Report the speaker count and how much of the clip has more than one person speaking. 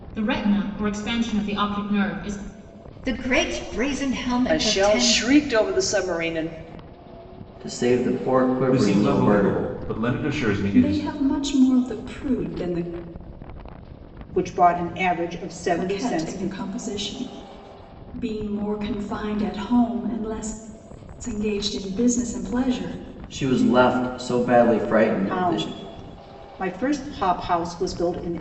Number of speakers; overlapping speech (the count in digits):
7, about 12%